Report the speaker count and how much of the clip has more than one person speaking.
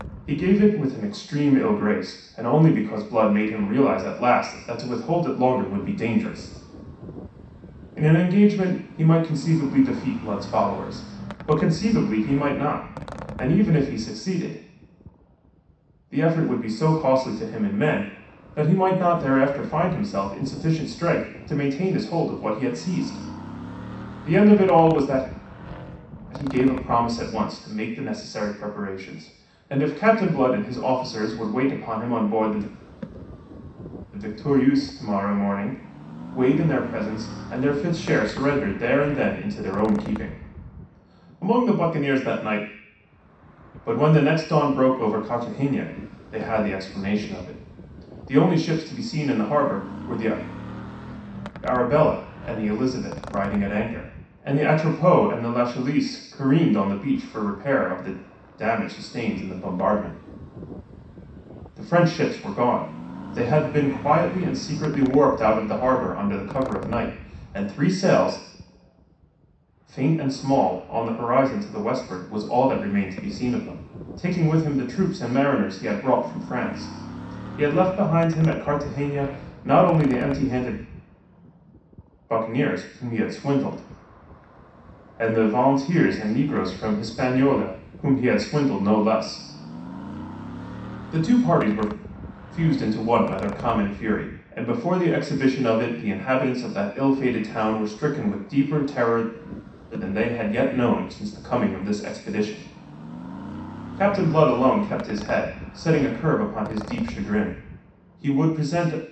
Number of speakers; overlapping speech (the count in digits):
1, no overlap